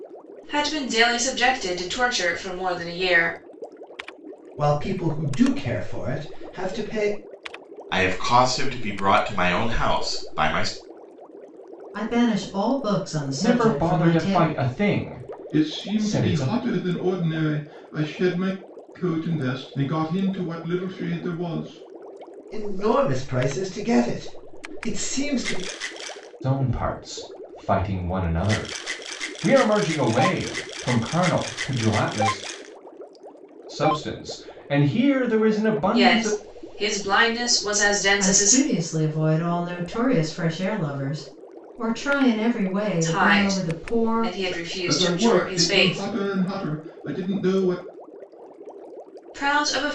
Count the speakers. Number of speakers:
6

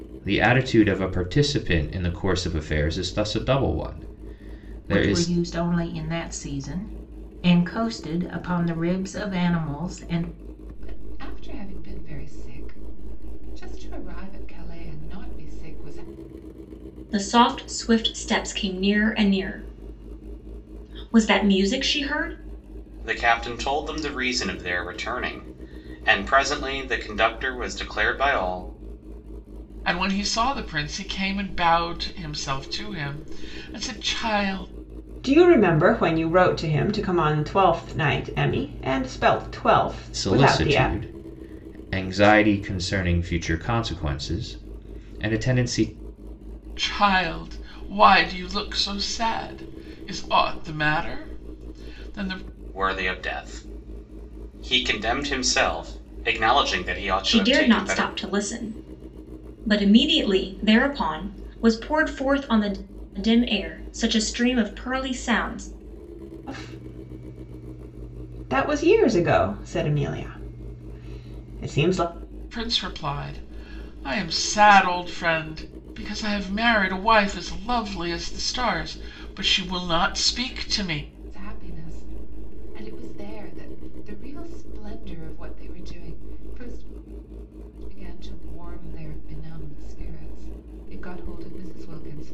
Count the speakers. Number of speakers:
7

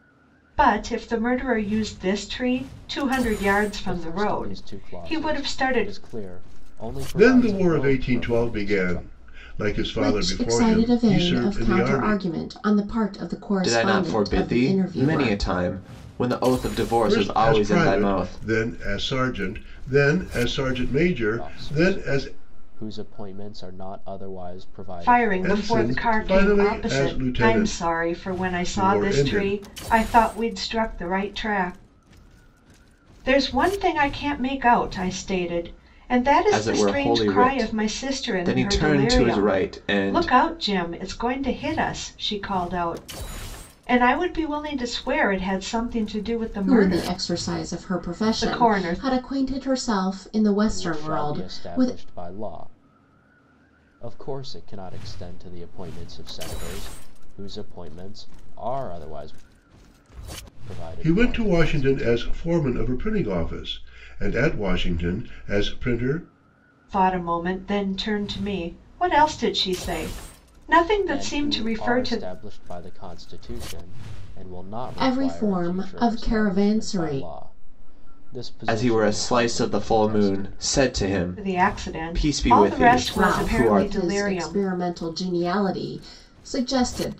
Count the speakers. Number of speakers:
5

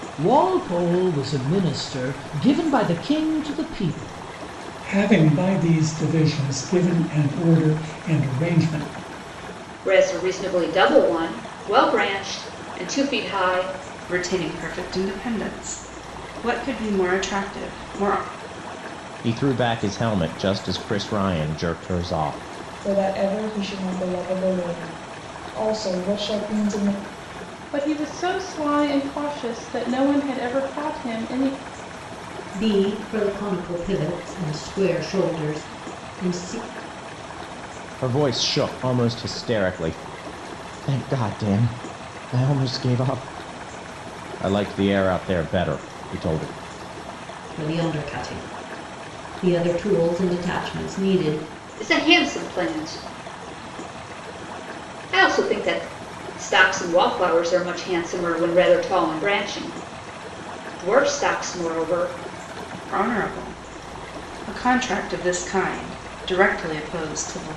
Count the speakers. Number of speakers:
8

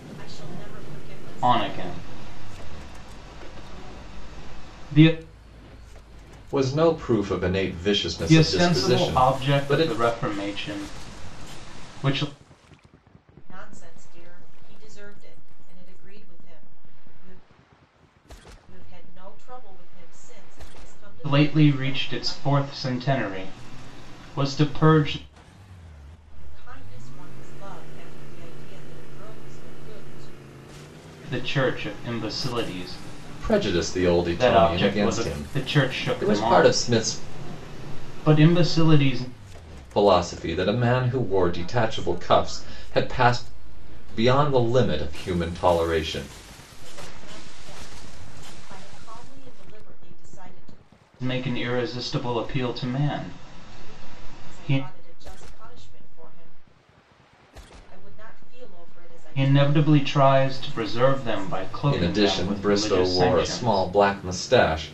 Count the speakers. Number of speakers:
3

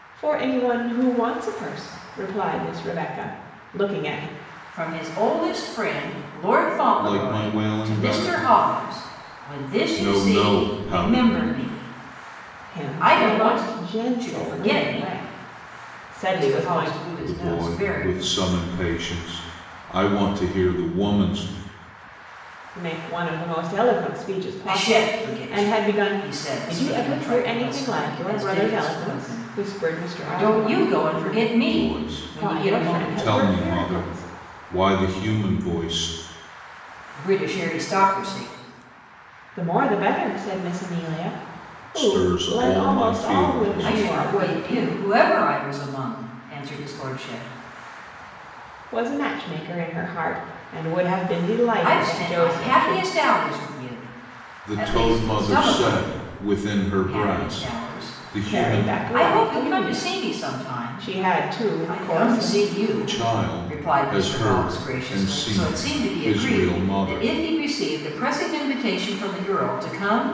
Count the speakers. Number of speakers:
3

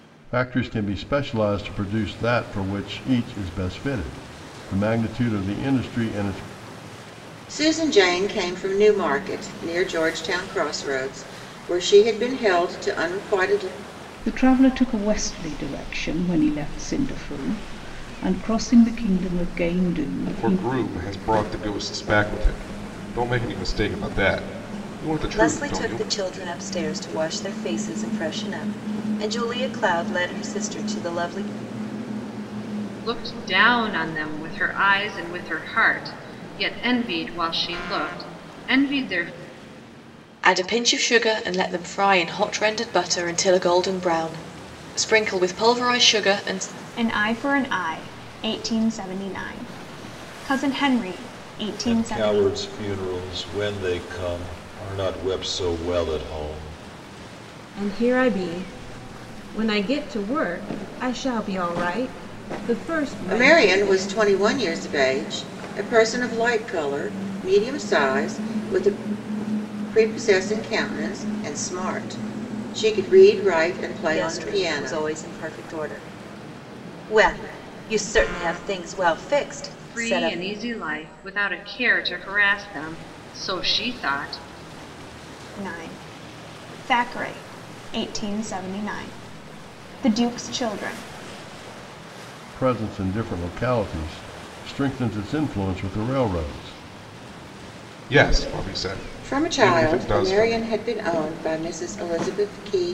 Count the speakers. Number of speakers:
10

